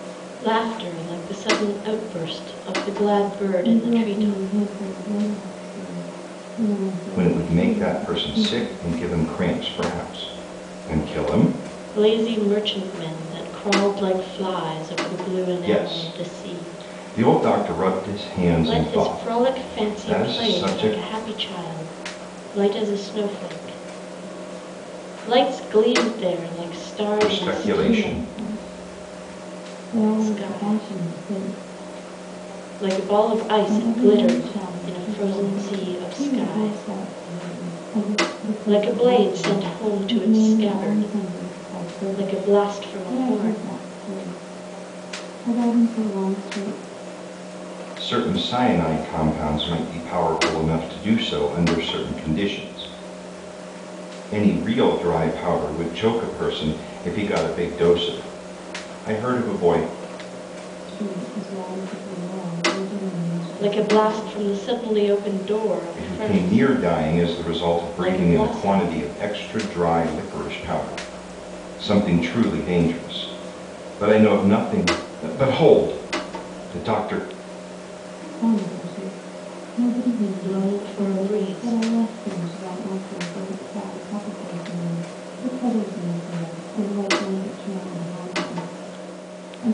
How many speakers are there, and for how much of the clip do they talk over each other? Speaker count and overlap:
three, about 25%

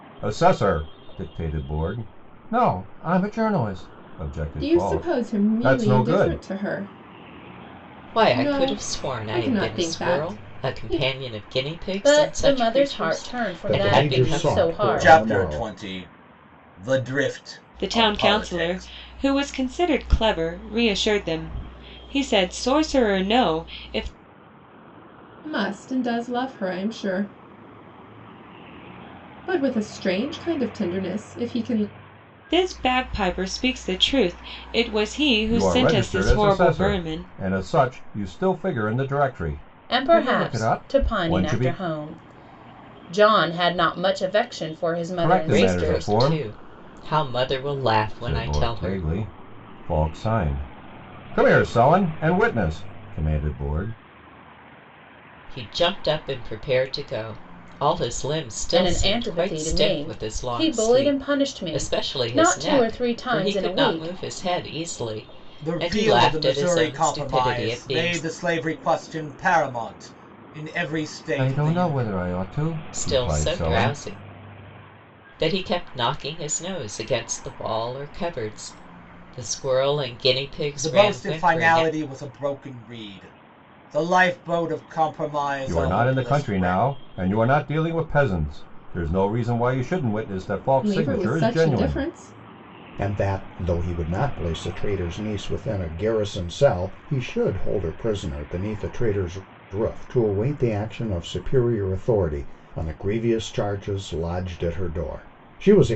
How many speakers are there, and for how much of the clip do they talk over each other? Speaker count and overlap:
seven, about 27%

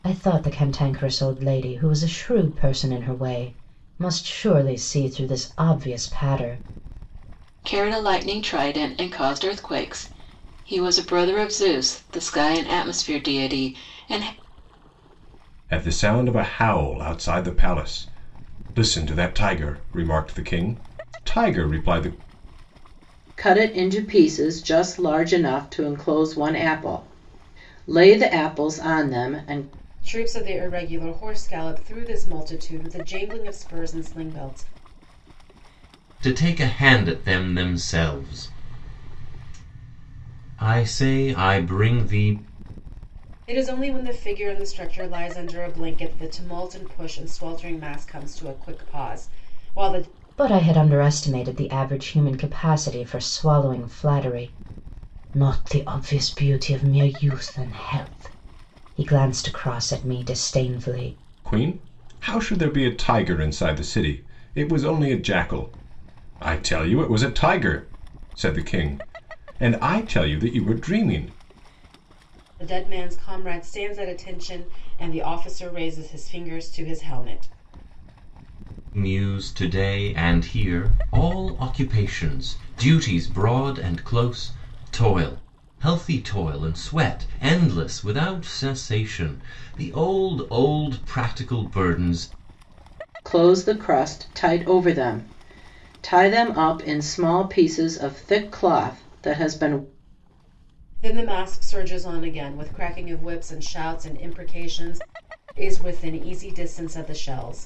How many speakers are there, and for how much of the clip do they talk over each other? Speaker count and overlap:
six, no overlap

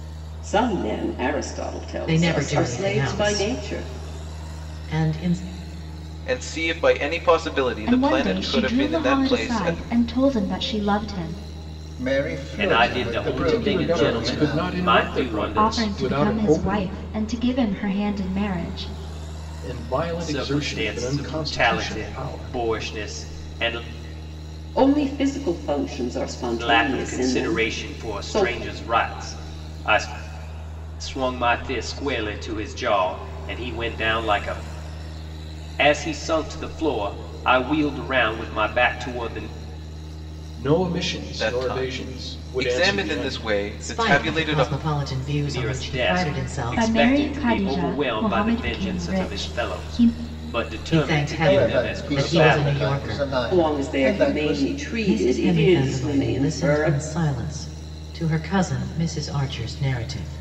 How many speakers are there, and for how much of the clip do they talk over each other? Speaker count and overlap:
seven, about 43%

